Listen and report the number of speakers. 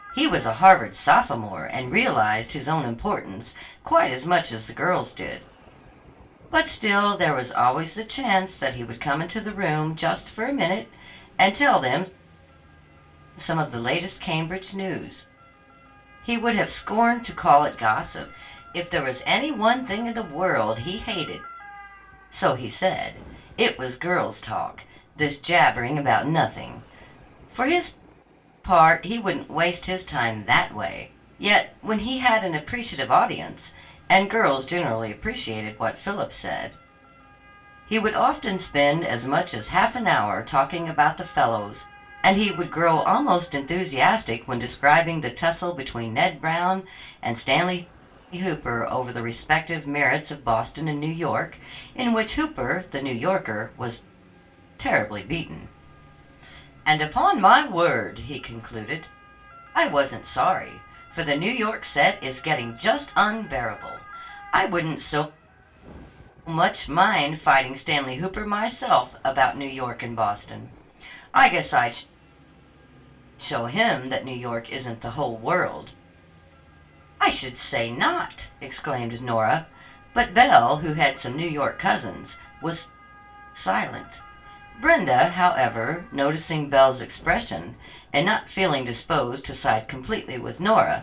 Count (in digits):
1